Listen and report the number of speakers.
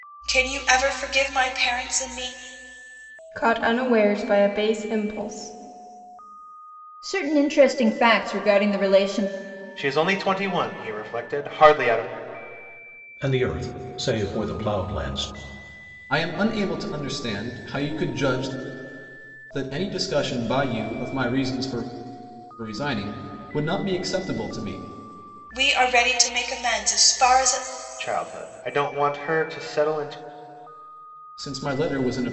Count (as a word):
six